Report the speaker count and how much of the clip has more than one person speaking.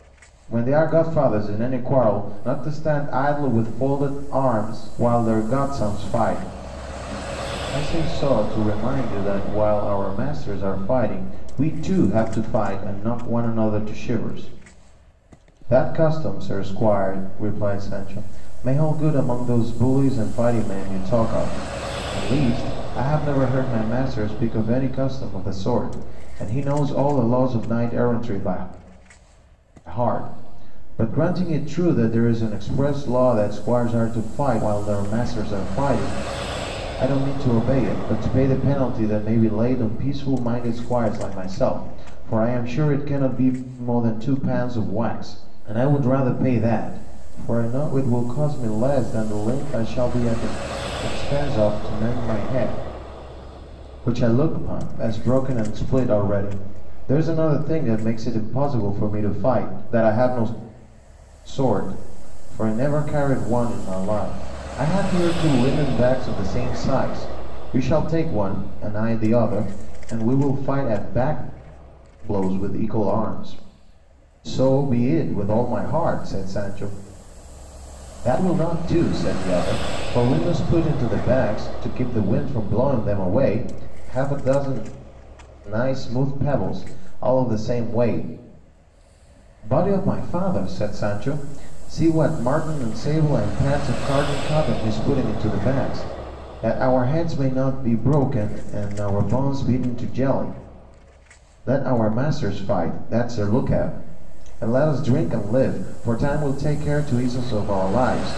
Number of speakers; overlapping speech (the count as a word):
one, no overlap